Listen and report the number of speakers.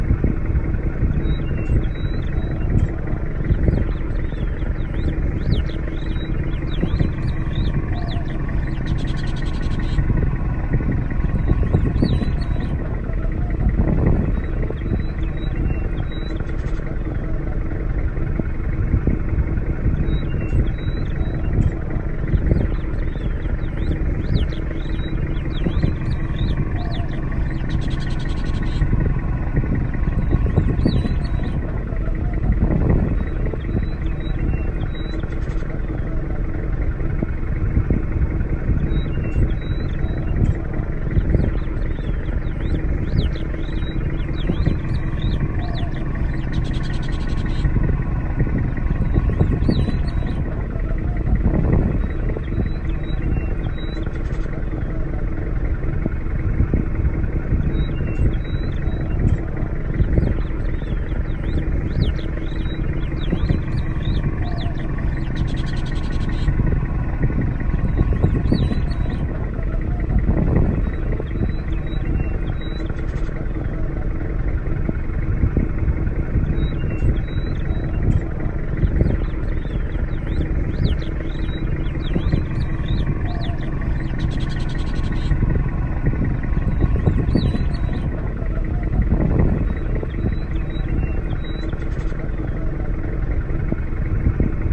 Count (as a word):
zero